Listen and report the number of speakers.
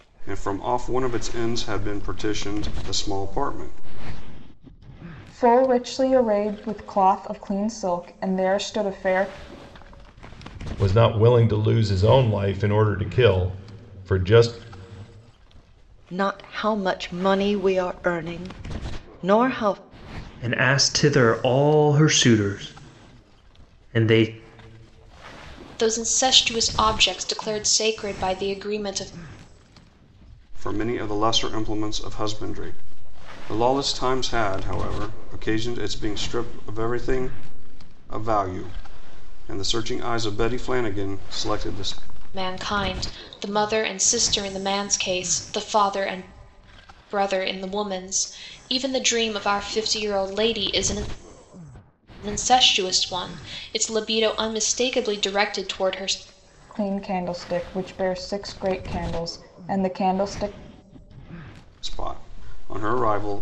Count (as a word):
six